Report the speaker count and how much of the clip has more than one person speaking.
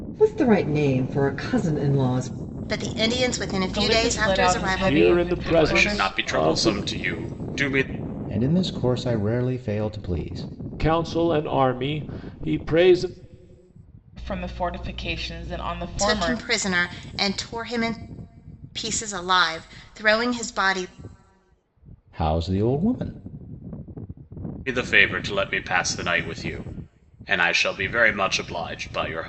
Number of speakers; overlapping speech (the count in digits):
6, about 12%